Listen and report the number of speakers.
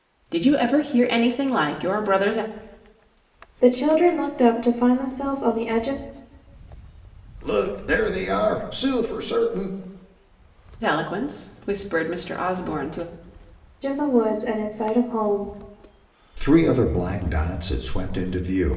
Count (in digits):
3